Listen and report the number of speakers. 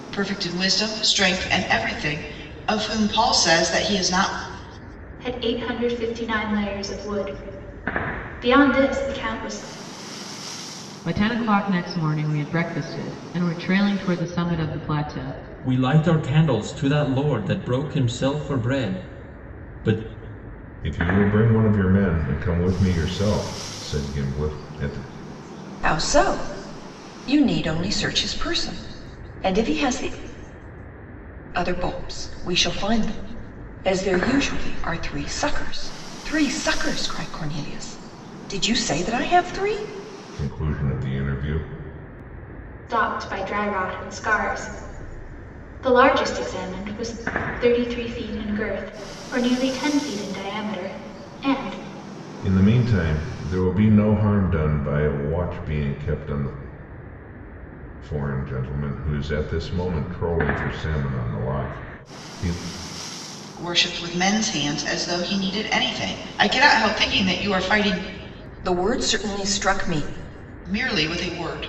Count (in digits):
6